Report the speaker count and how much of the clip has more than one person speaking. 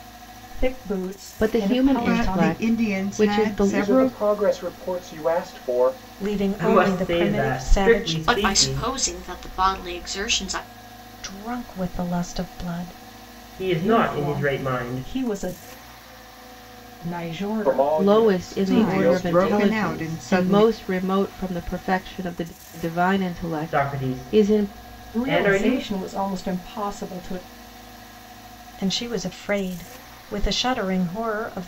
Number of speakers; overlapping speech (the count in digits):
7, about 36%